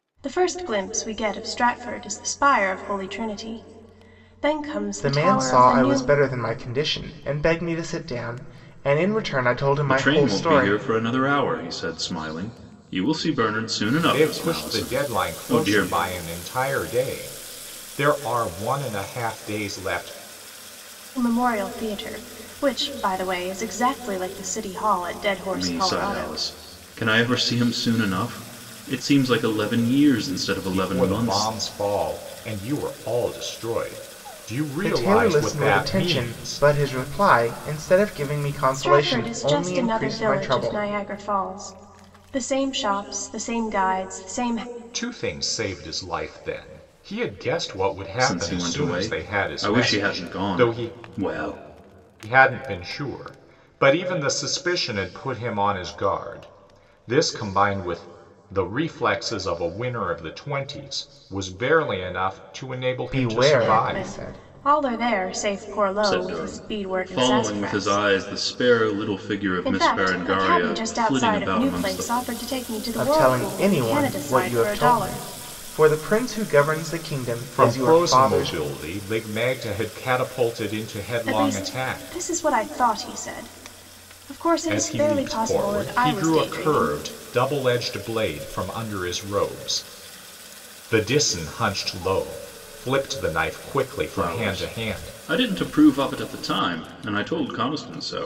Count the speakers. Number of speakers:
4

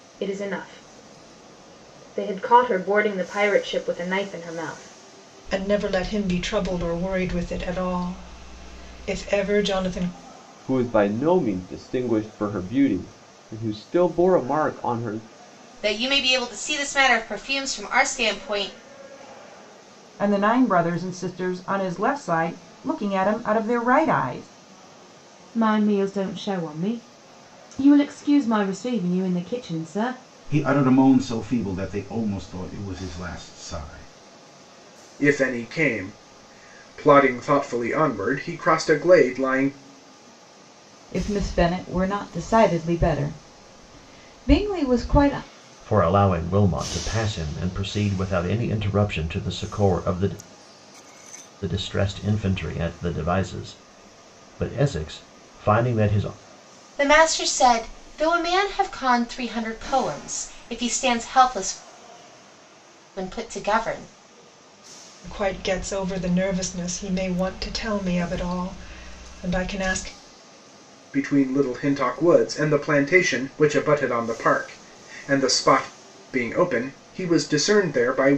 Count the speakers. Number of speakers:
10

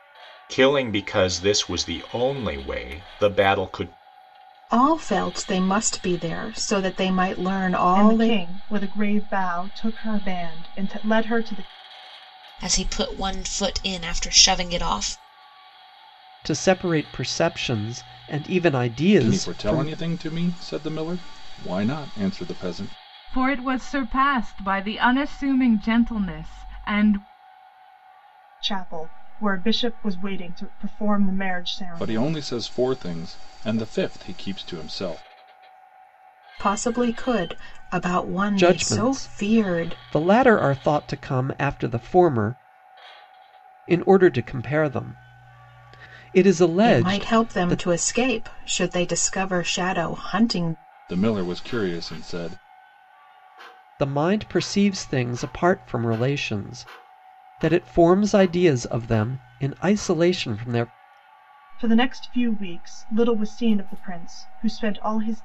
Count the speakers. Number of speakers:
7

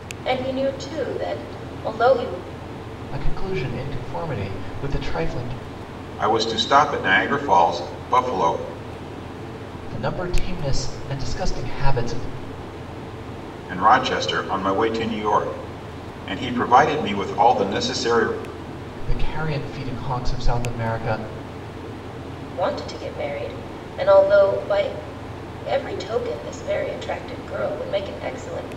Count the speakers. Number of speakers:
3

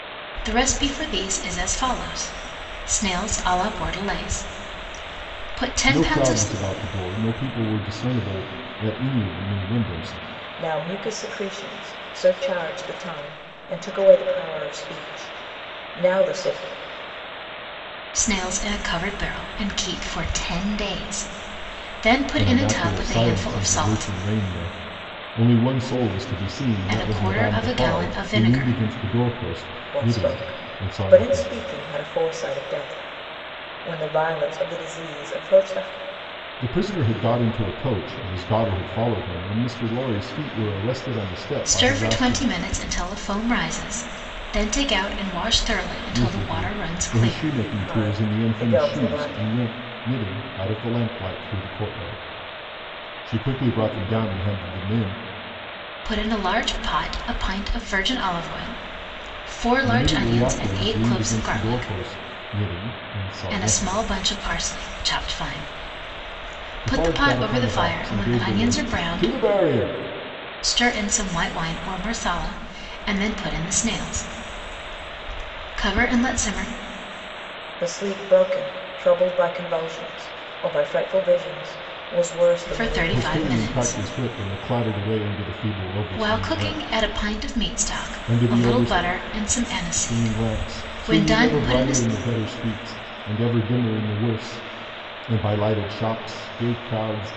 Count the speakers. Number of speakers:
3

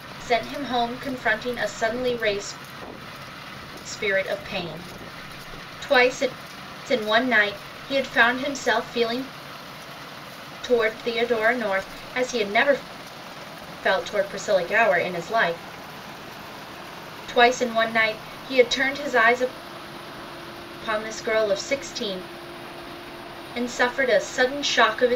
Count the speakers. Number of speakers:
1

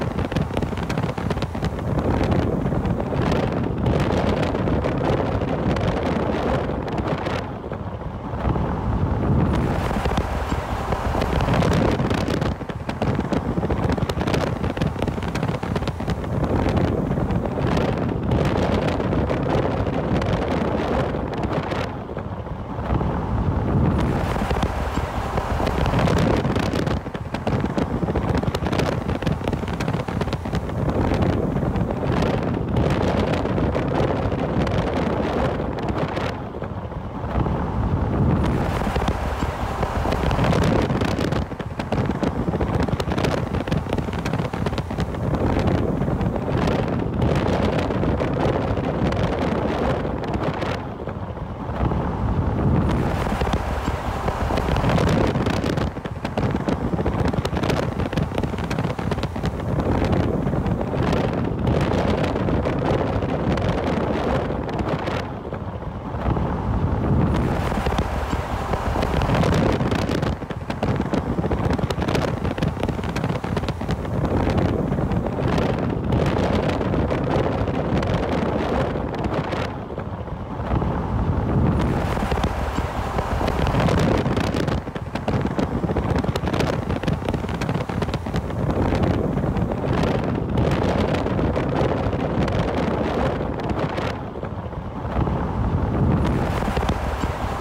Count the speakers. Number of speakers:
0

